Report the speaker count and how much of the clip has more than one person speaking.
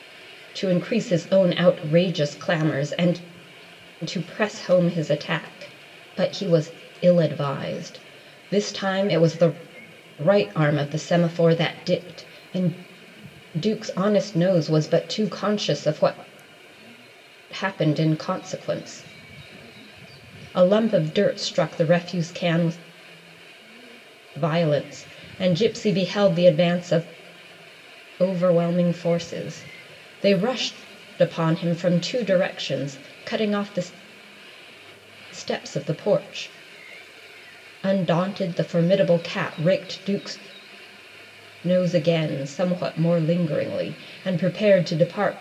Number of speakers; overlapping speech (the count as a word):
one, no overlap